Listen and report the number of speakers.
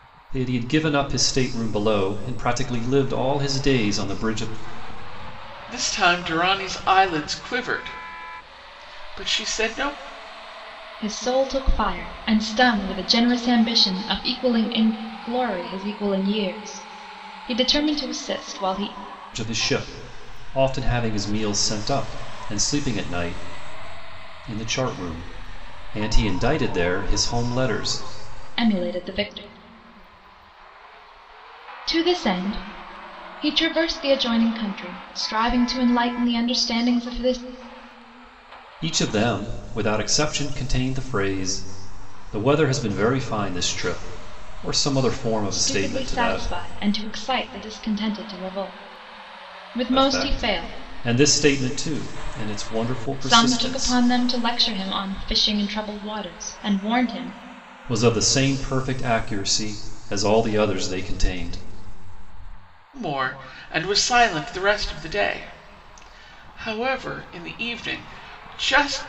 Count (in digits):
3